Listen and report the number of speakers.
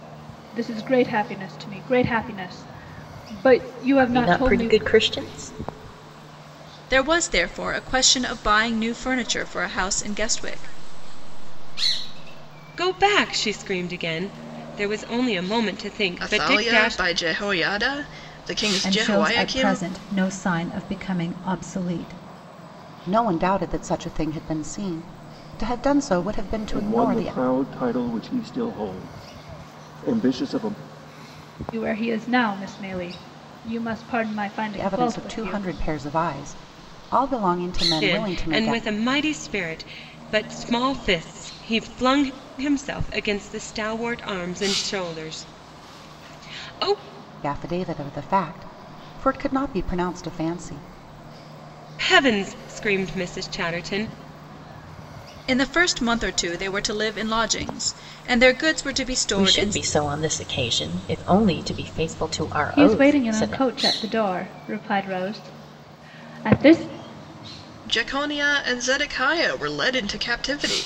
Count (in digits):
9